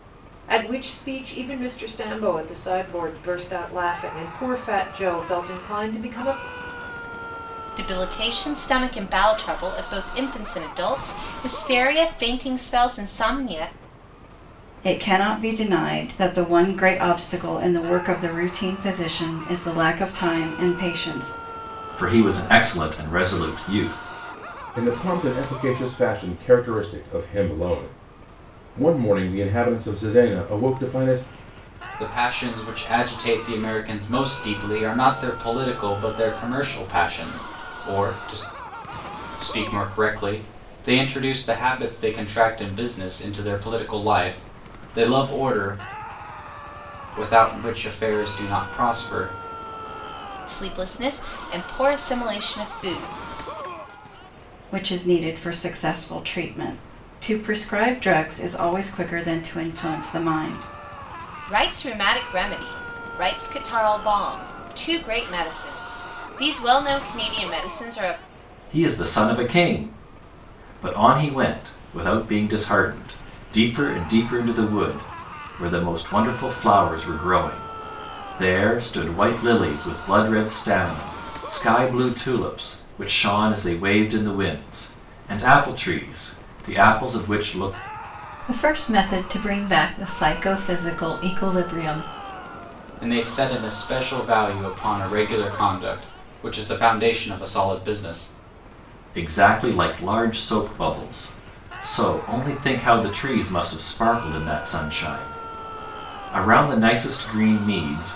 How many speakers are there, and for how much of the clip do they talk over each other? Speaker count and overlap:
6, no overlap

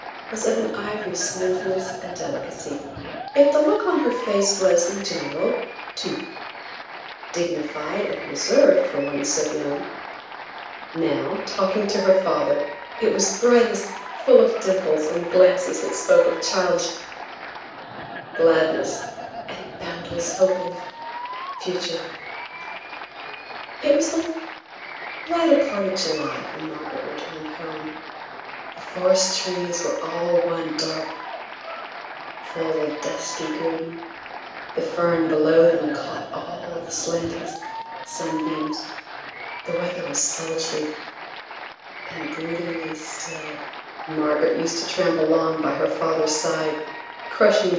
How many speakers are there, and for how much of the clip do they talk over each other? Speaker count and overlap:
1, no overlap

